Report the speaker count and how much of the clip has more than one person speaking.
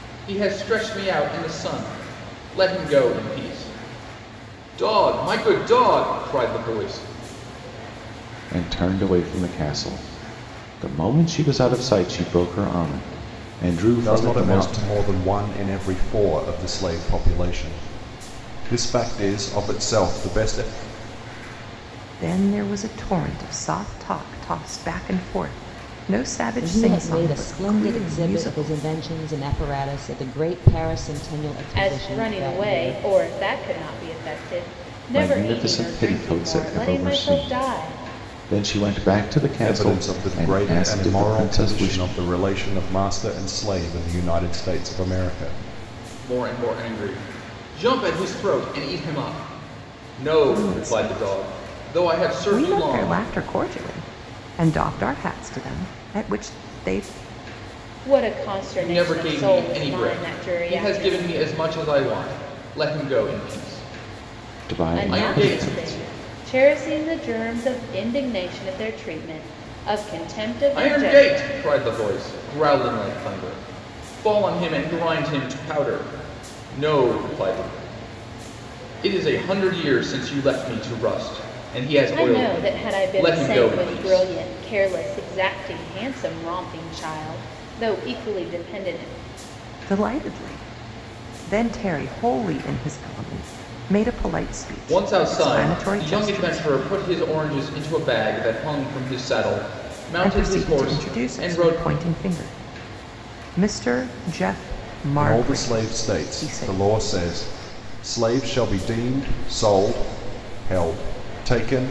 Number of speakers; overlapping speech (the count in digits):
6, about 22%